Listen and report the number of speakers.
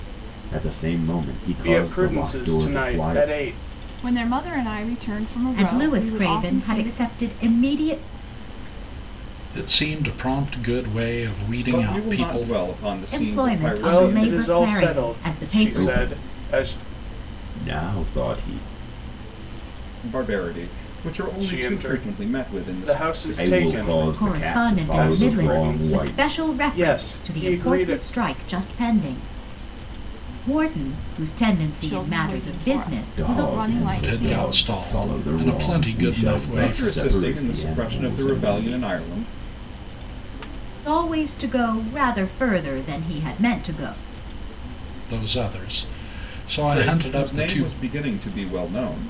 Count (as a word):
six